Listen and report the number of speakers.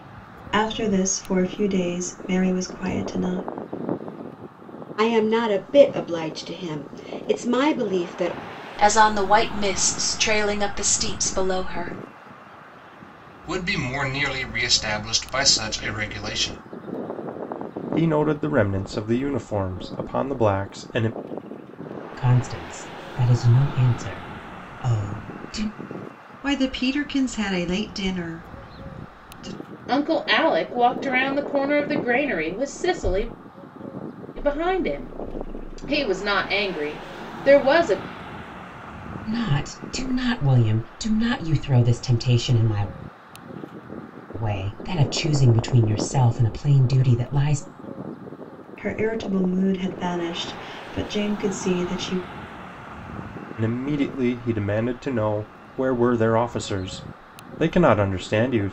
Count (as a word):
eight